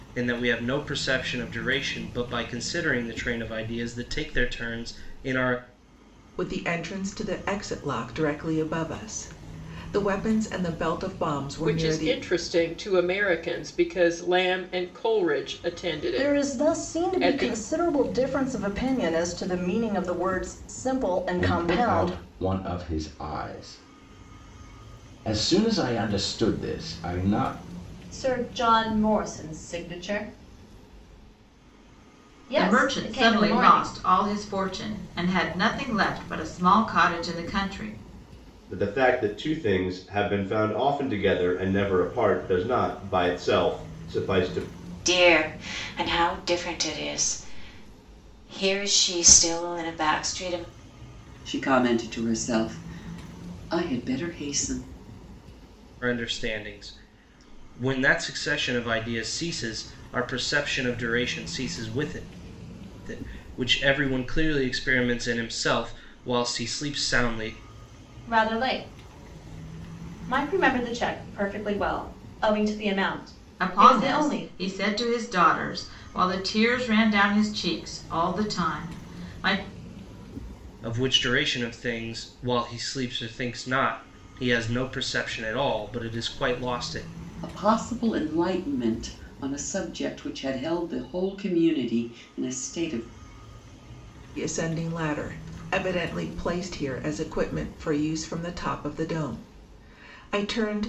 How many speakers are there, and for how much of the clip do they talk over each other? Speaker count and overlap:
ten, about 5%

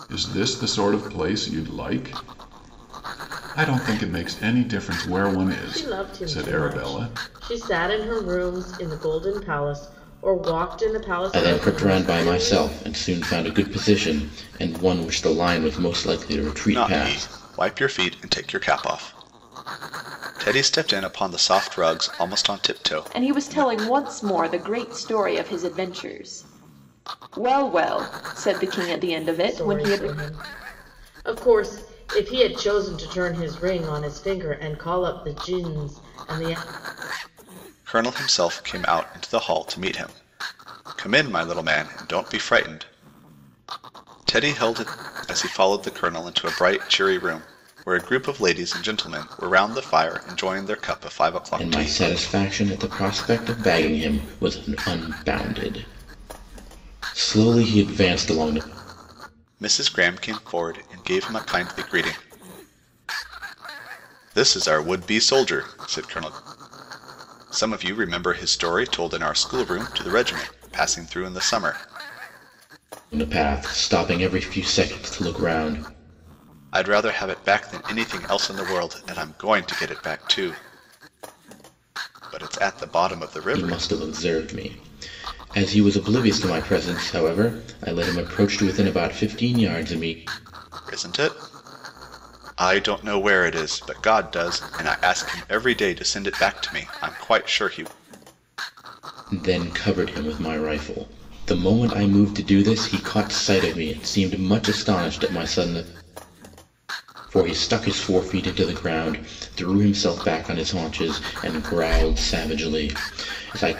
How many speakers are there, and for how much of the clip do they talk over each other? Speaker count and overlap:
five, about 5%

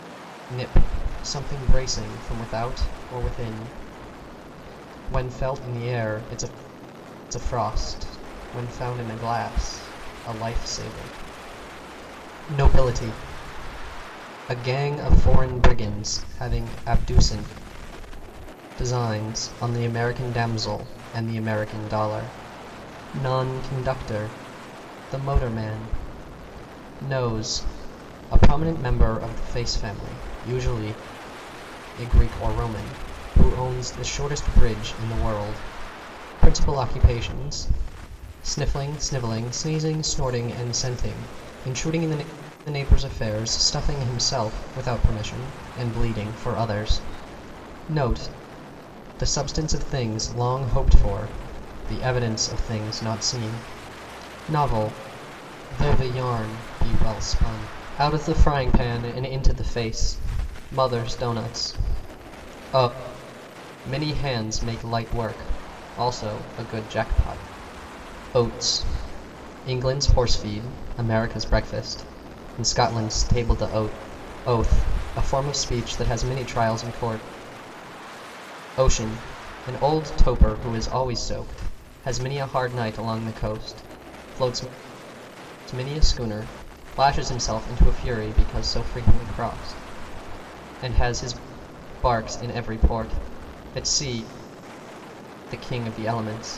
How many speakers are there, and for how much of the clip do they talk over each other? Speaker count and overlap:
one, no overlap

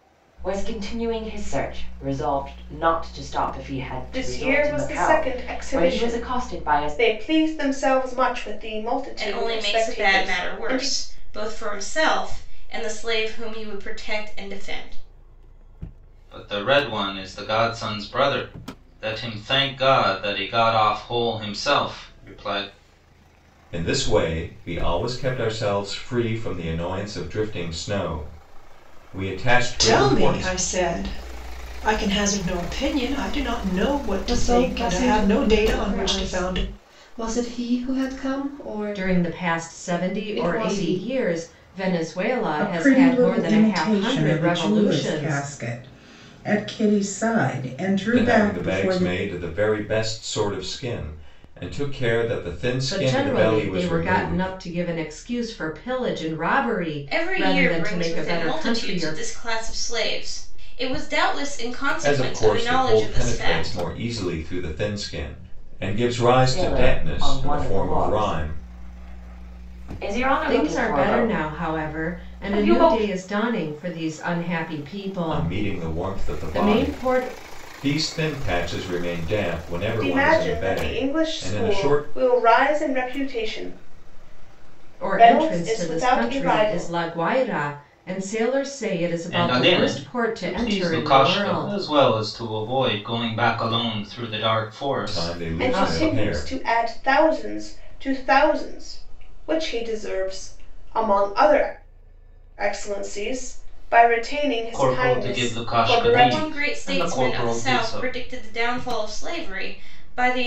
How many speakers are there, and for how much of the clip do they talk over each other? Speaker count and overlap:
nine, about 35%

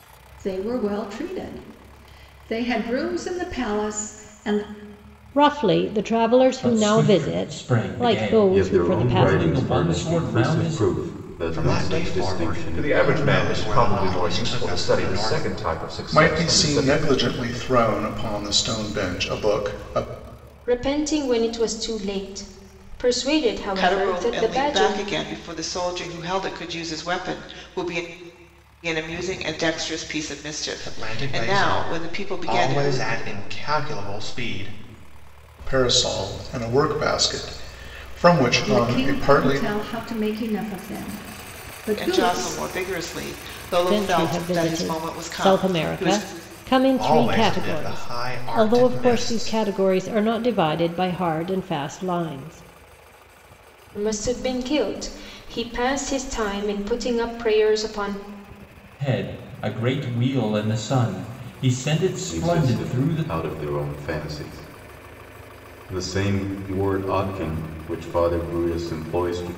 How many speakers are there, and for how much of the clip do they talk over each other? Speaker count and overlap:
nine, about 29%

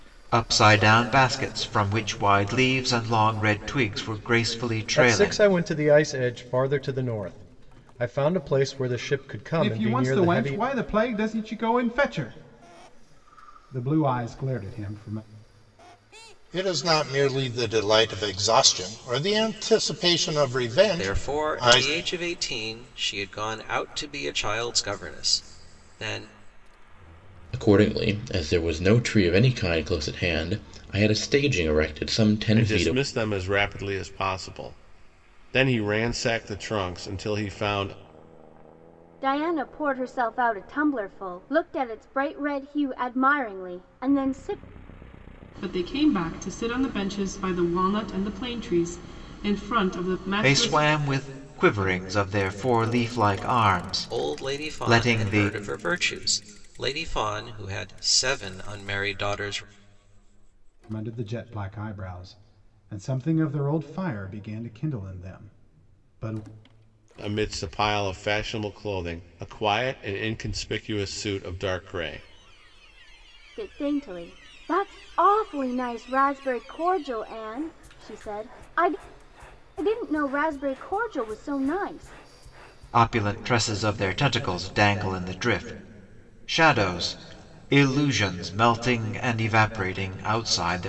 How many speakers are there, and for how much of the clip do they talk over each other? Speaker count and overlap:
nine, about 5%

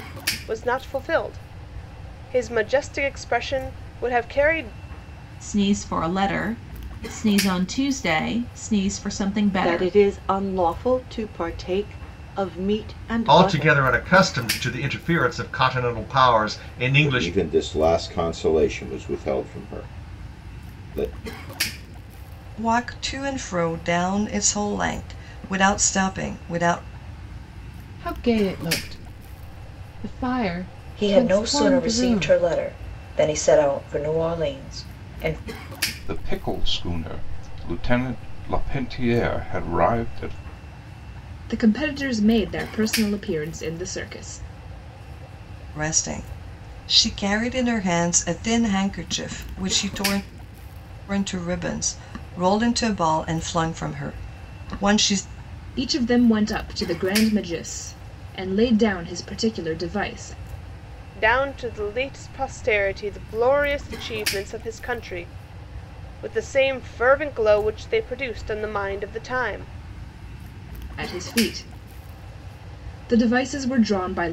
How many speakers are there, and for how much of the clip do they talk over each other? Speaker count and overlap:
ten, about 4%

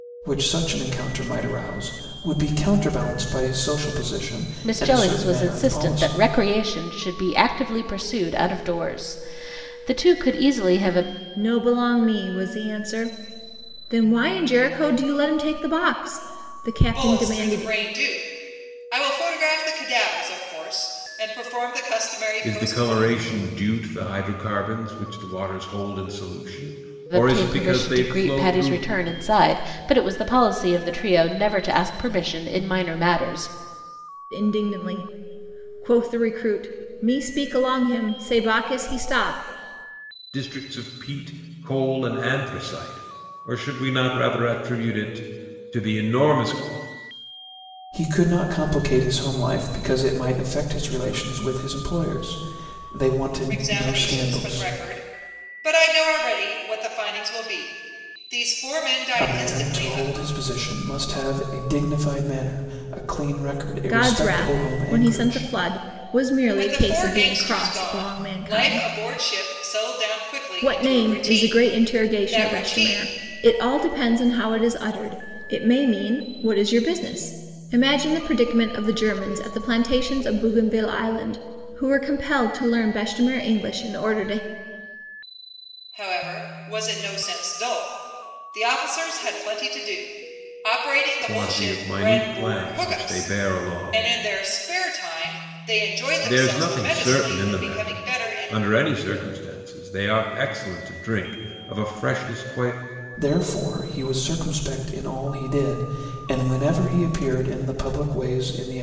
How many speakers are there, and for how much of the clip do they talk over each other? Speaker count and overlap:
five, about 18%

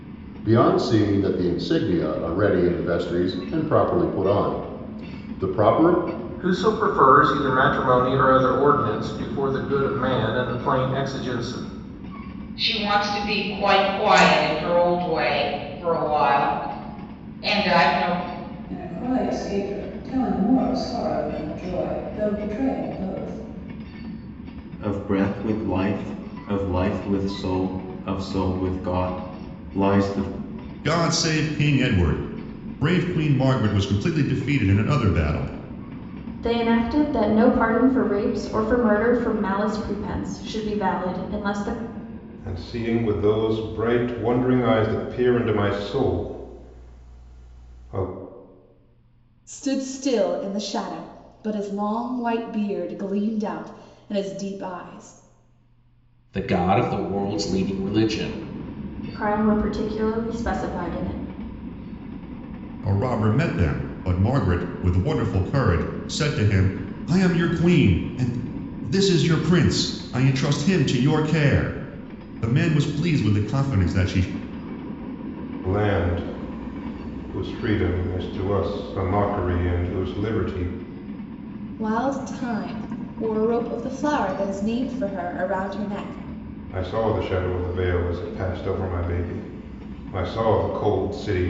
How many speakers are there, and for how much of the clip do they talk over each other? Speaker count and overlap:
ten, no overlap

